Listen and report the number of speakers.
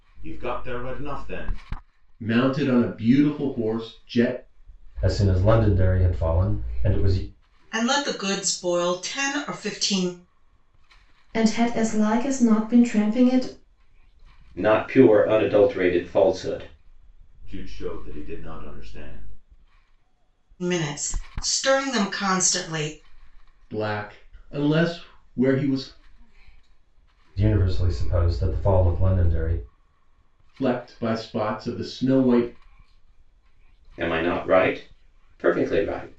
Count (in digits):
6